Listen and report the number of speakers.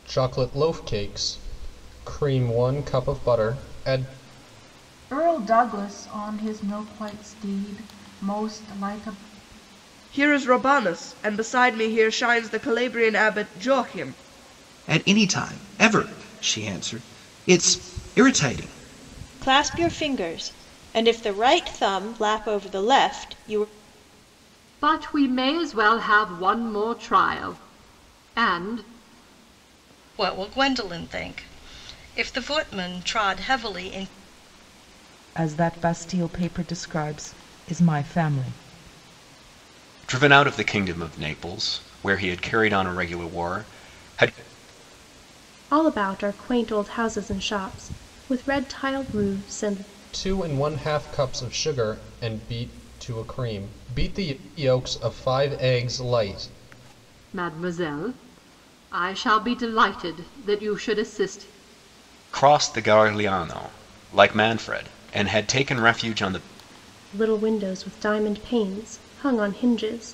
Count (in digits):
10